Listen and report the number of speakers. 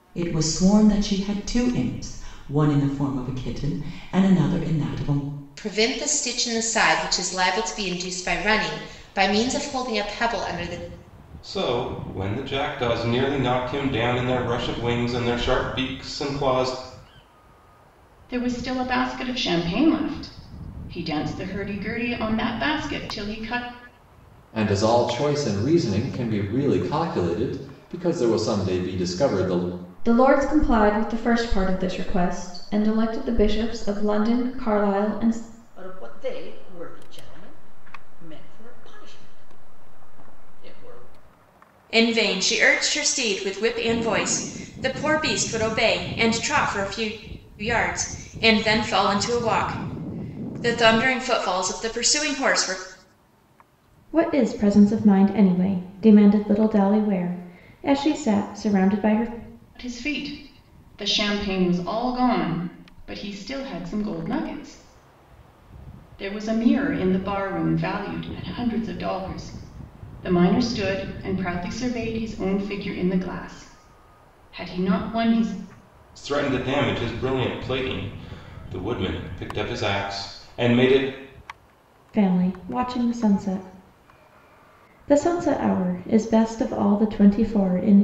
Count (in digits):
8